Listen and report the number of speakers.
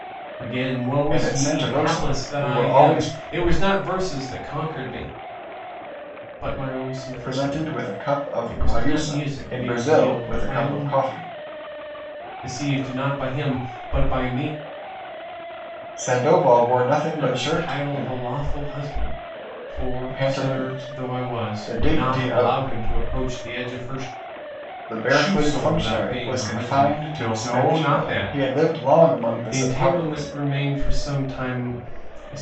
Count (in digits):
2